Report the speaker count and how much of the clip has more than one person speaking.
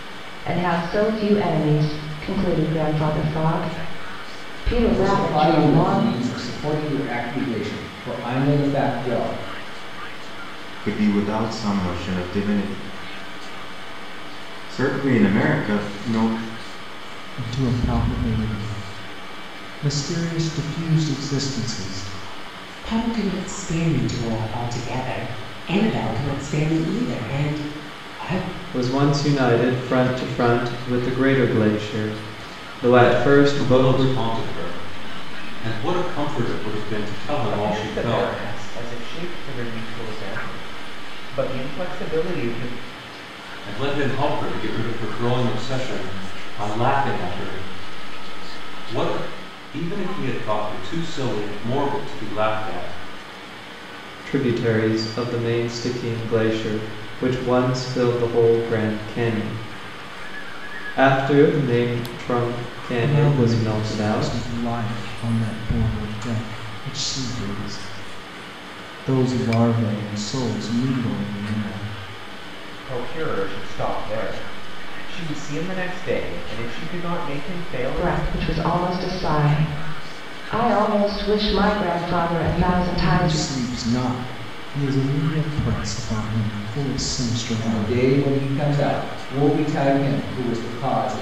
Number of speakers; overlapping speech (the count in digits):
8, about 7%